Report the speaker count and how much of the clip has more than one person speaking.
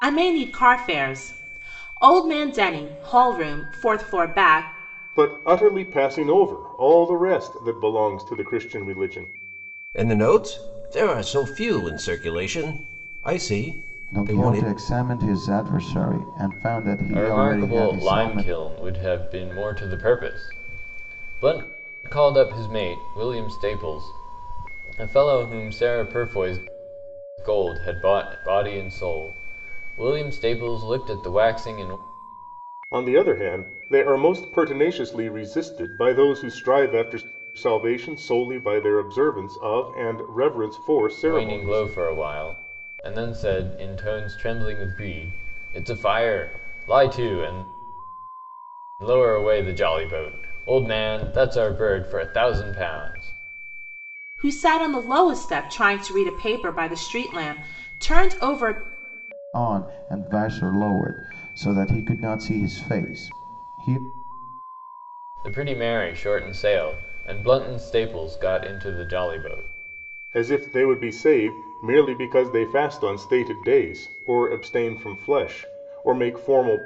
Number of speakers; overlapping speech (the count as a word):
five, about 4%